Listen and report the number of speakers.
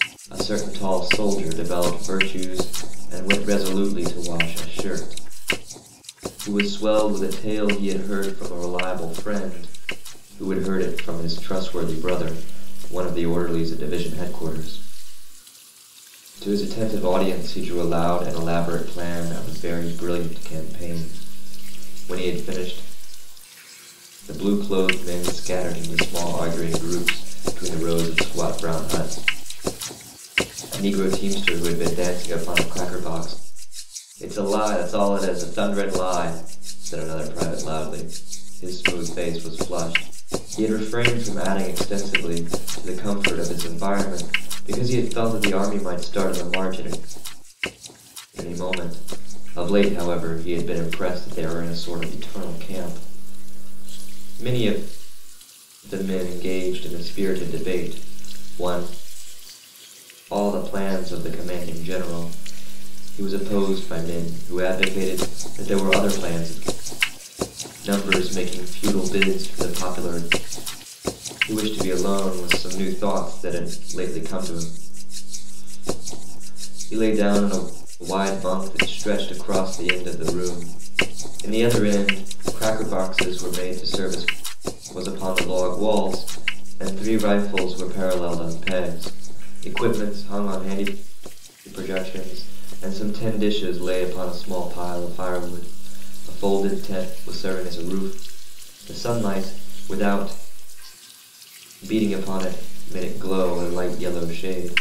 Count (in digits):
1